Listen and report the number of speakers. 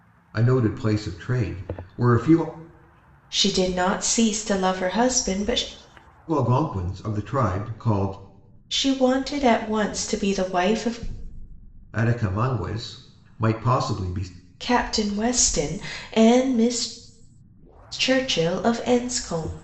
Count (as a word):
two